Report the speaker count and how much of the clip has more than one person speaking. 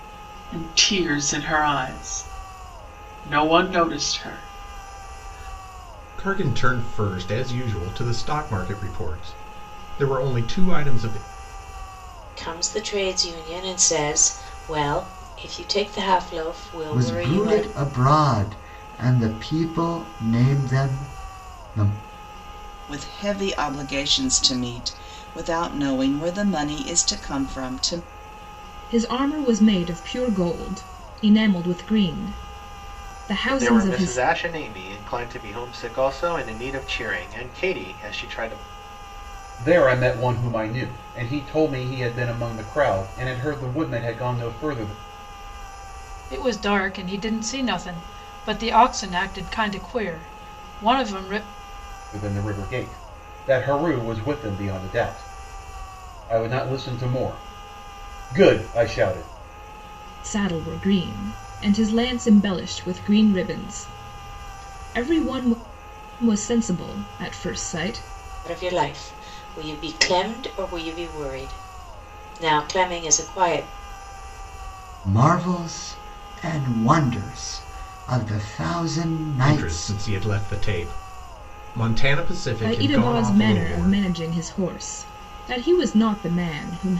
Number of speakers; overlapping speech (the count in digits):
9, about 4%